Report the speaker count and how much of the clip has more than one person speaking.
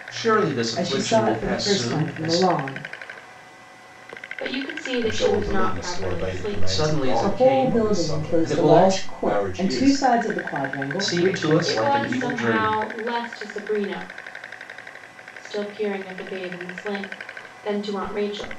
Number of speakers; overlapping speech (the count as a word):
four, about 46%